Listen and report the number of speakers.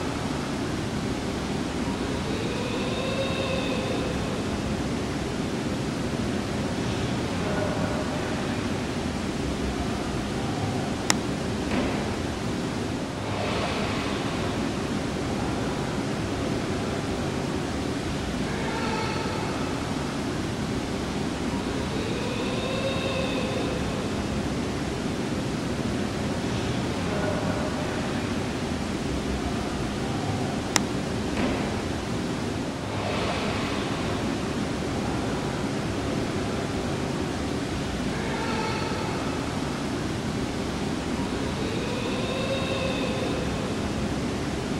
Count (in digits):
0